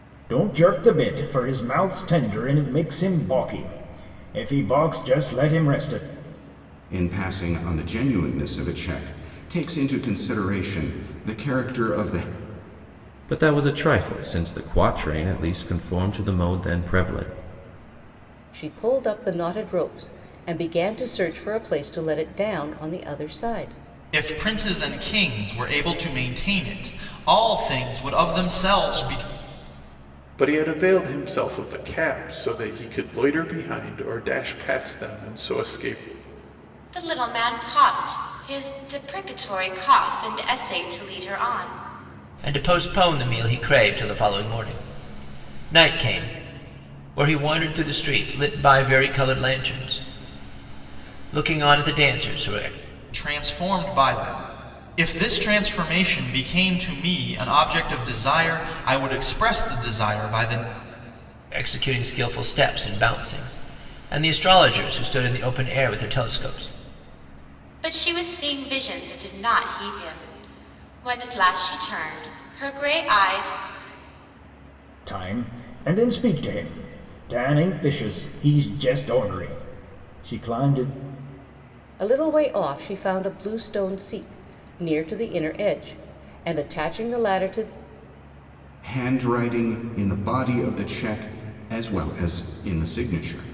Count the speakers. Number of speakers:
eight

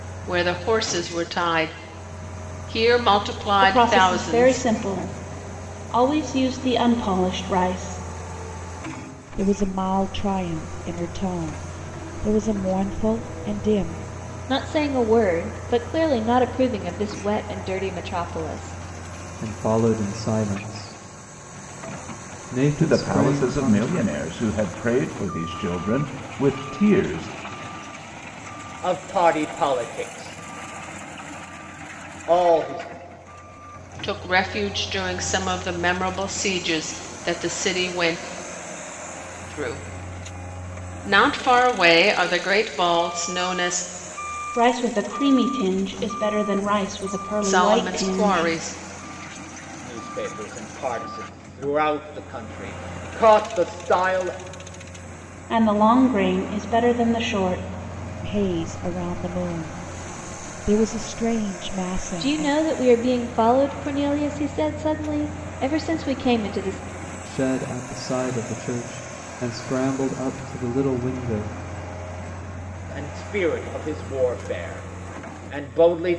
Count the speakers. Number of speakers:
seven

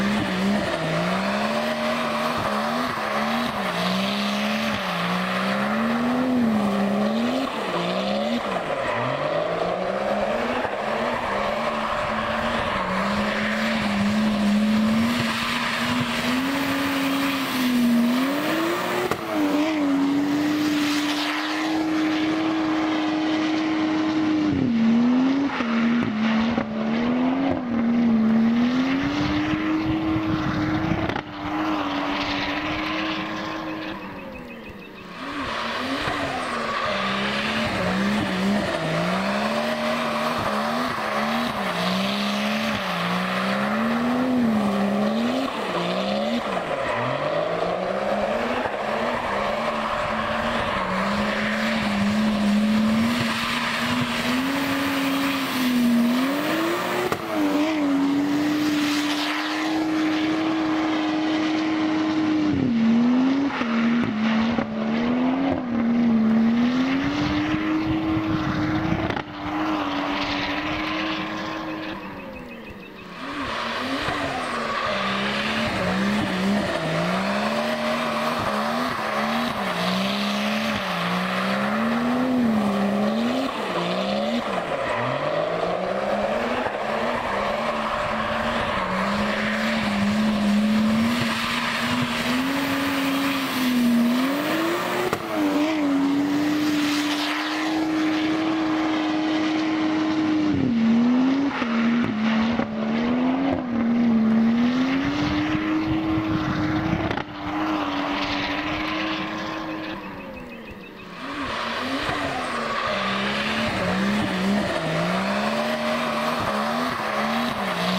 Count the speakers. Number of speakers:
zero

